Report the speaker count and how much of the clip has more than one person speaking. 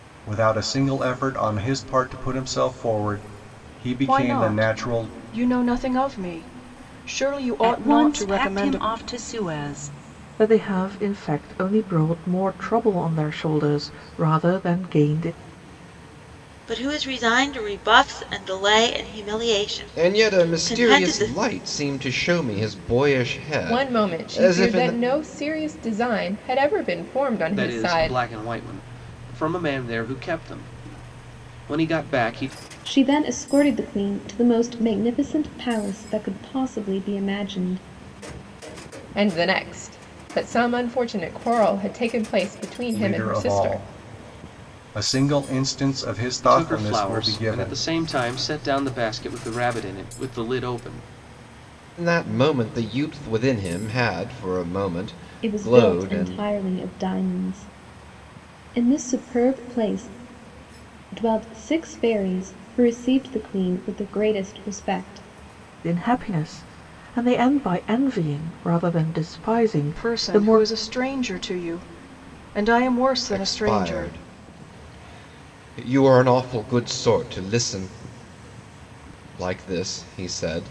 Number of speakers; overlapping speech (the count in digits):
9, about 13%